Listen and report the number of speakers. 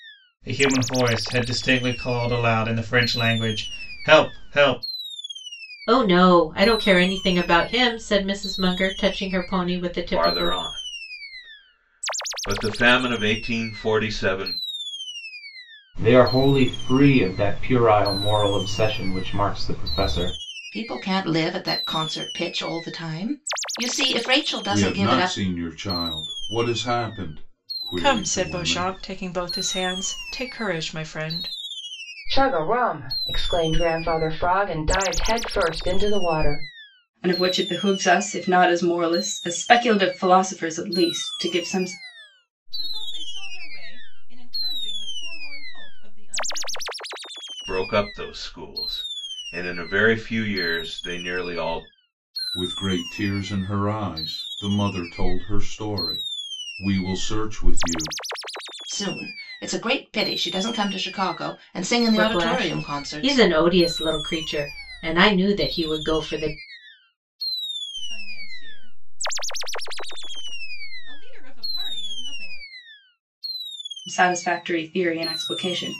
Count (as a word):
ten